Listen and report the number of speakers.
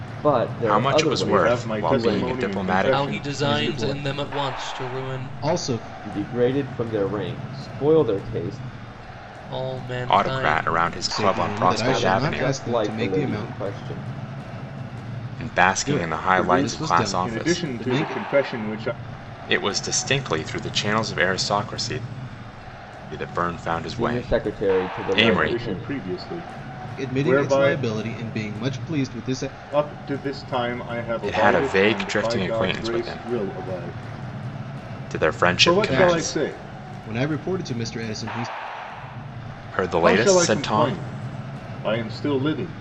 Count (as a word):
five